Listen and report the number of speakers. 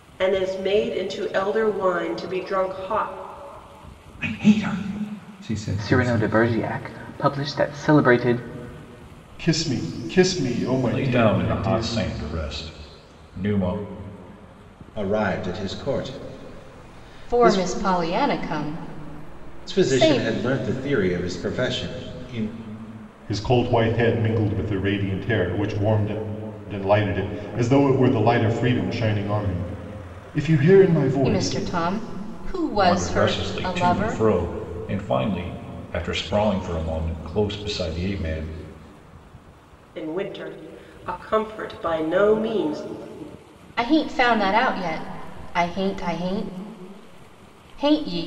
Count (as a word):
seven